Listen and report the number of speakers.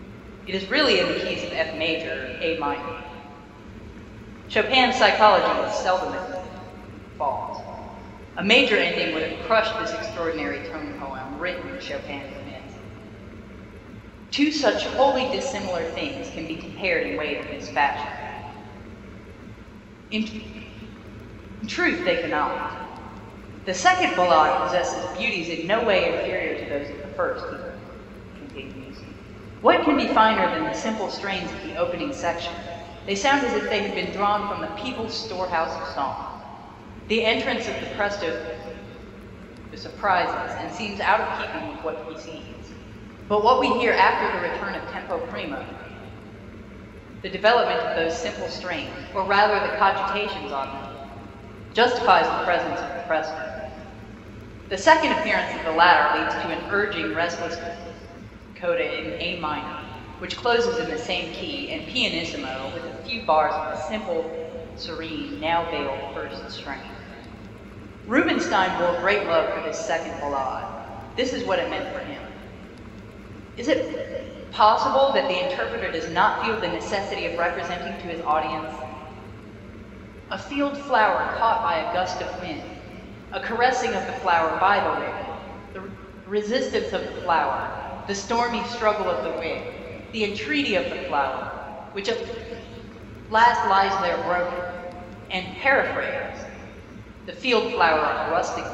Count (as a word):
one